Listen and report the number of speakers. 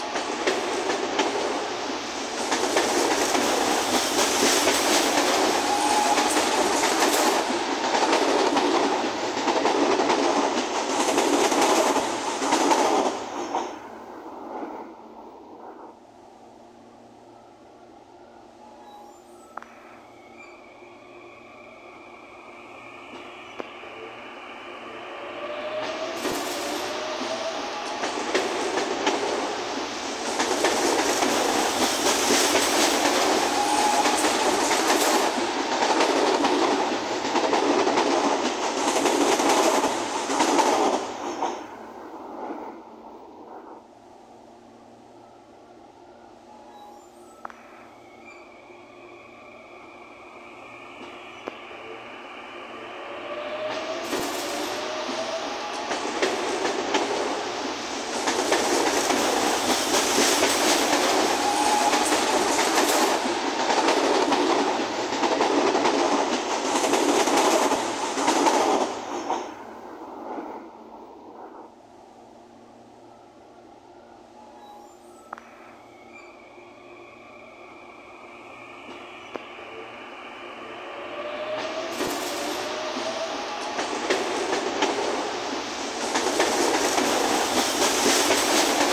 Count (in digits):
0